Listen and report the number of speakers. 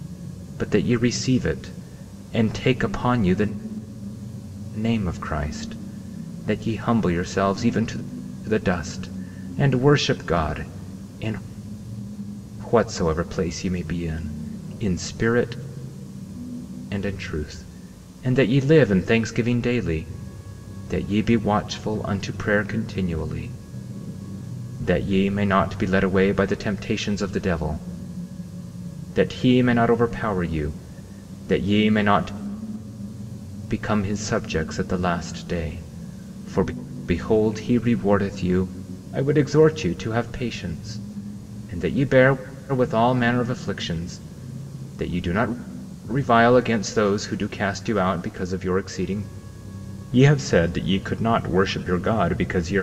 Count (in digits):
1